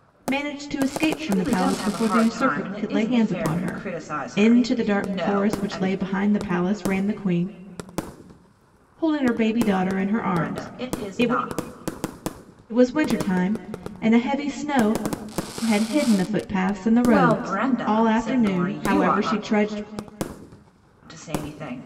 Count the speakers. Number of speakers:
2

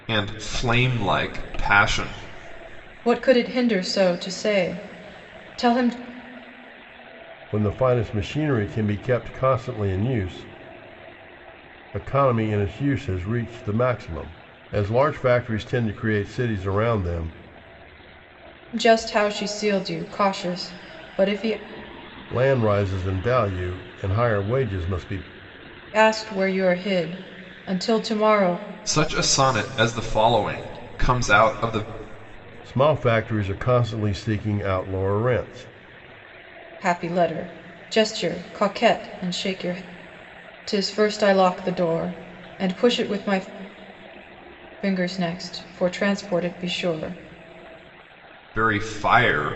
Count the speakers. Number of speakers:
3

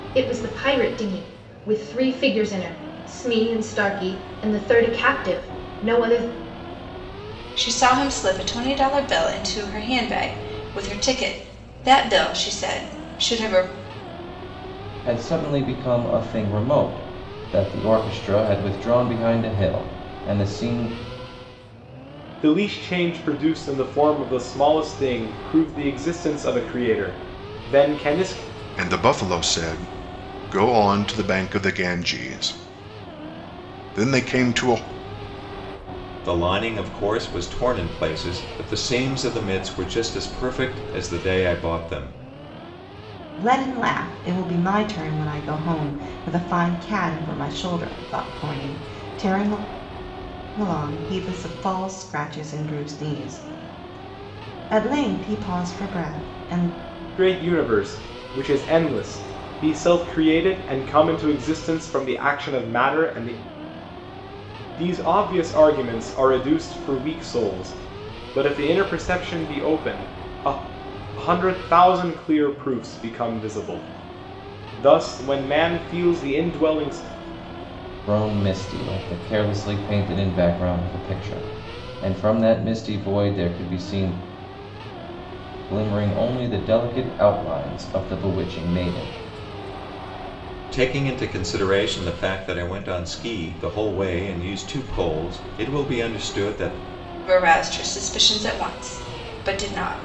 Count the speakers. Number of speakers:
7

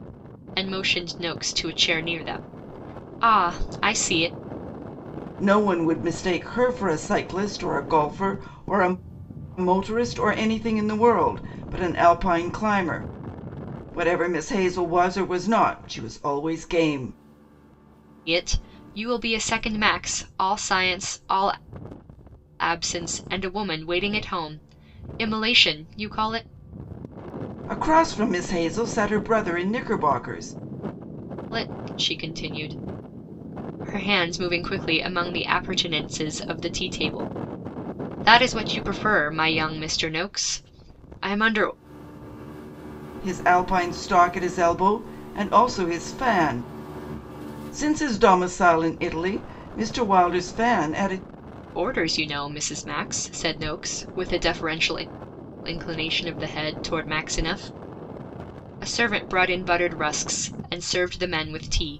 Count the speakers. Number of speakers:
2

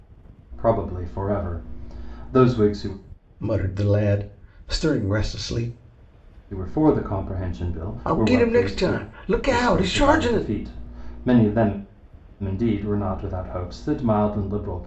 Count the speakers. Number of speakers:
2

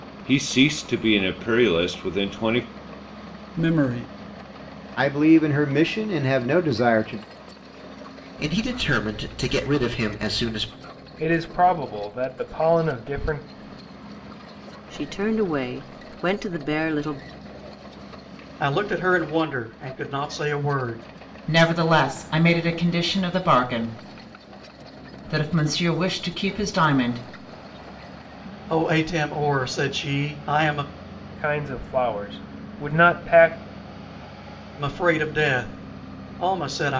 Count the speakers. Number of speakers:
8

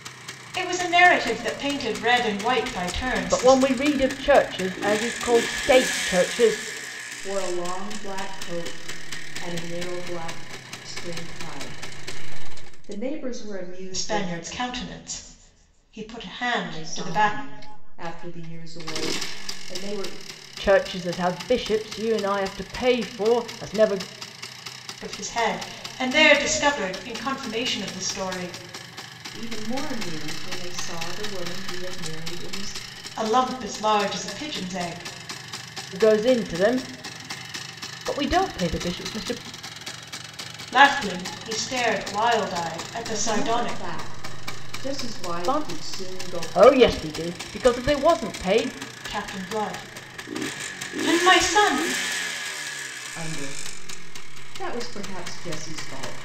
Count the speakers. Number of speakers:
3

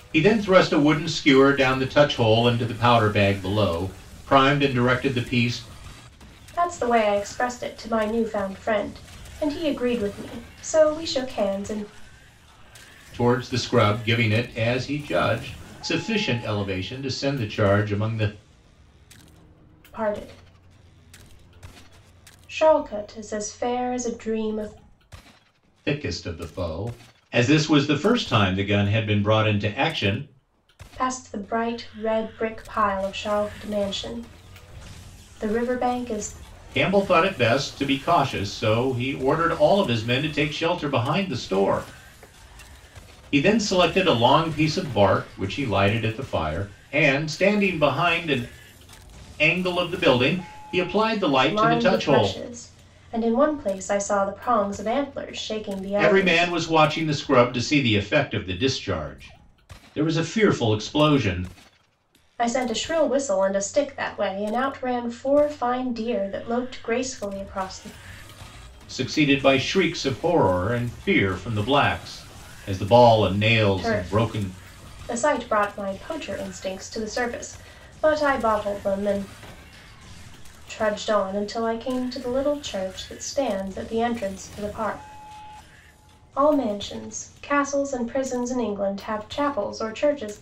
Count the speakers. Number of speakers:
2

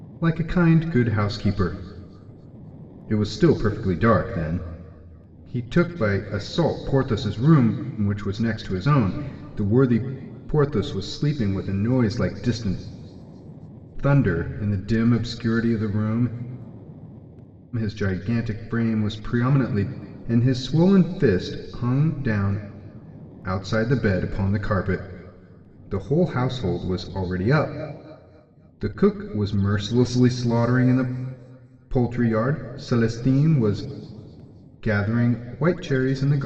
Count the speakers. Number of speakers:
1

